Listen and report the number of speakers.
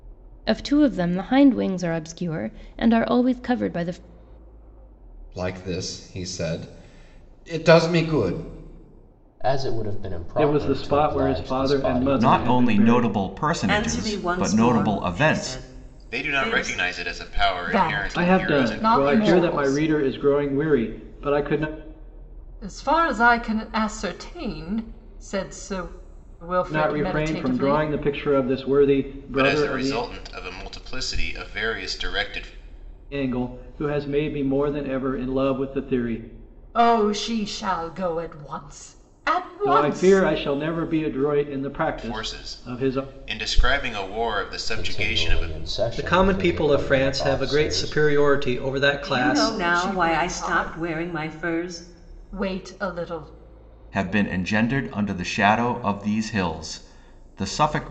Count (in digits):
8